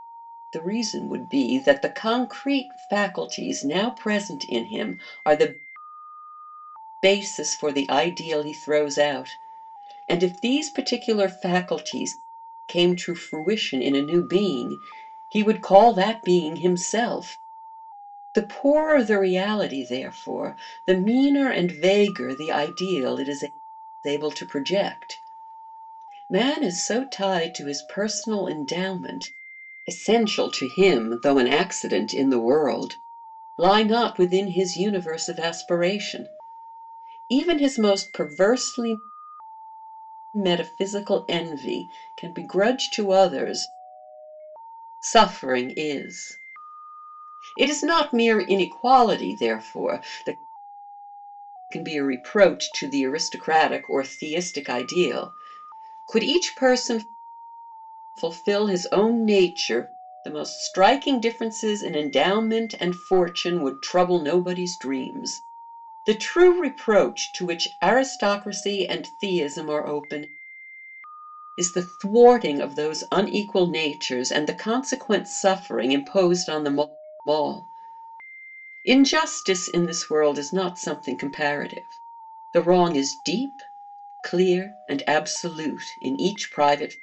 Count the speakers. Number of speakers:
1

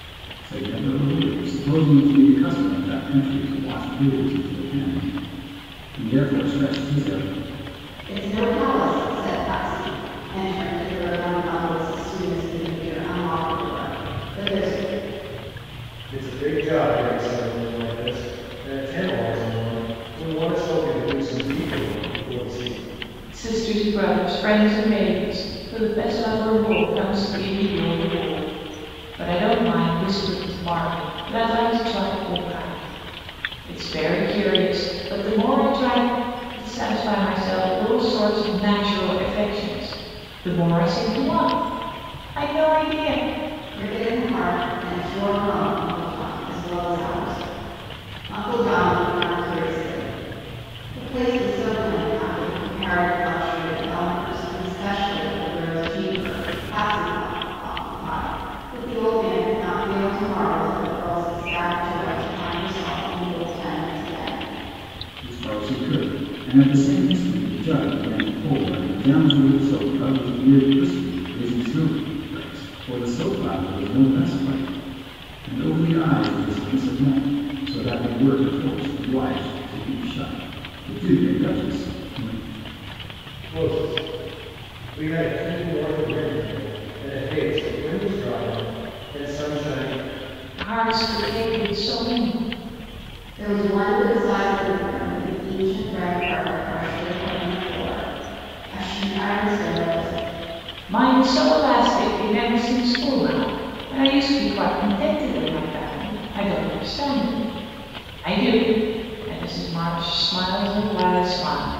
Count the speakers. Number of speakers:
4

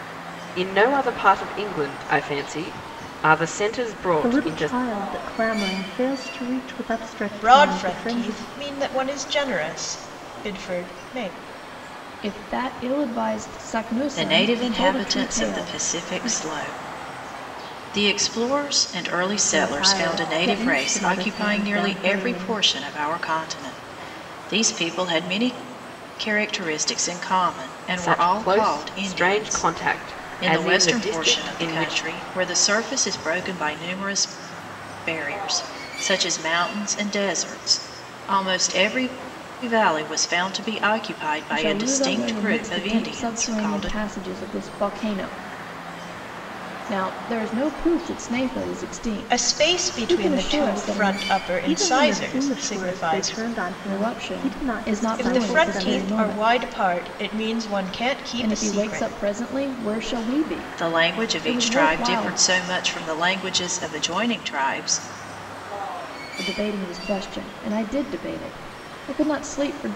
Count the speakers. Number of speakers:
5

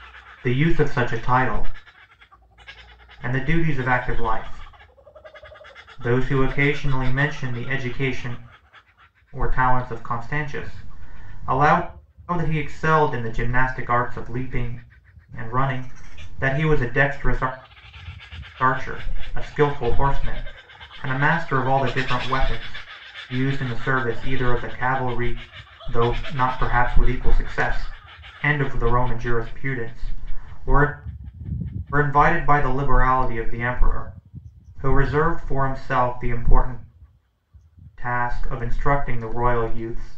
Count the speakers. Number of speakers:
1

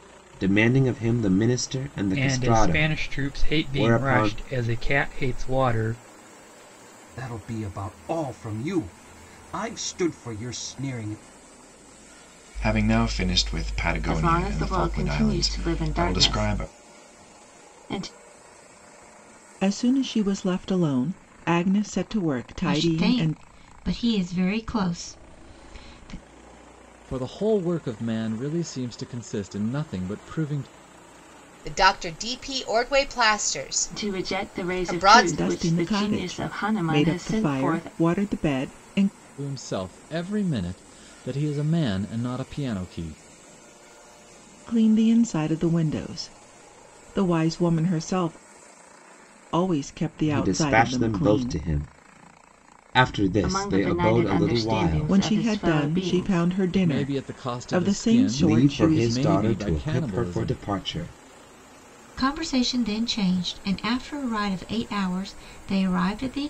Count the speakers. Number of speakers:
9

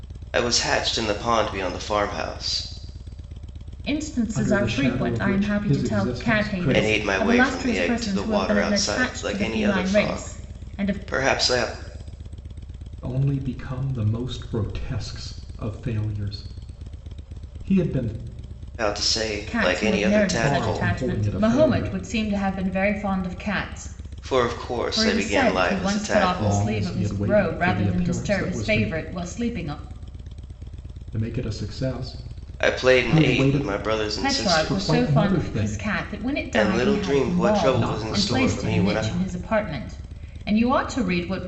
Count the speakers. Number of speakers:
3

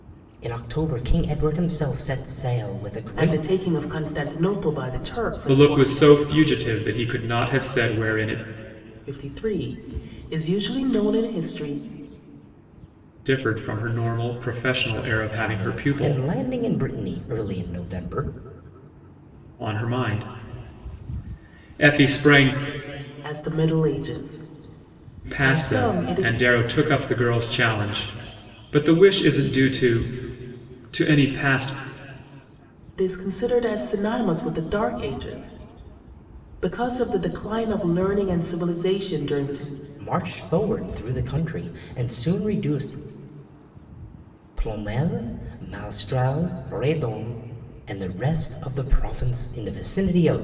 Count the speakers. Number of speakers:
3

